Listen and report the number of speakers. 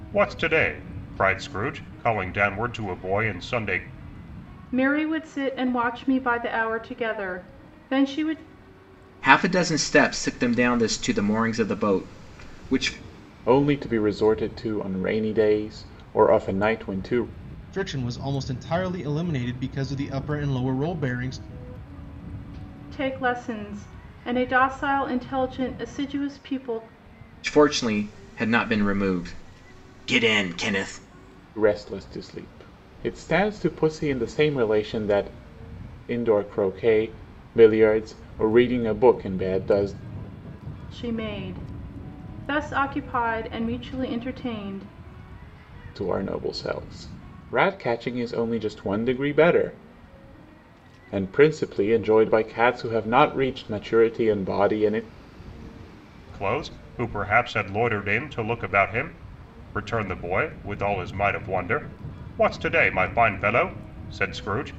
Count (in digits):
5